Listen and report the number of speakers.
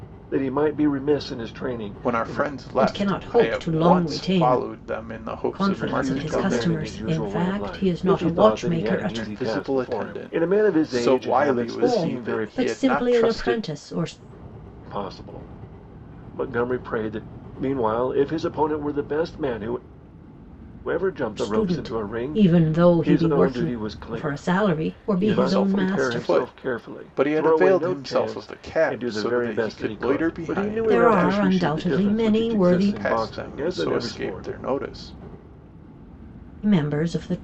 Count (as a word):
three